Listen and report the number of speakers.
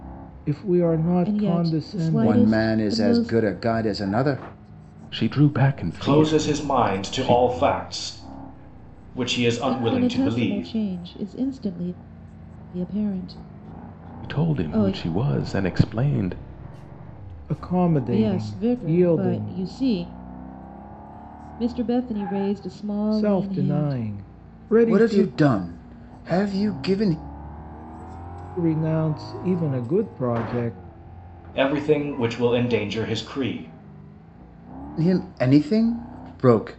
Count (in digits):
5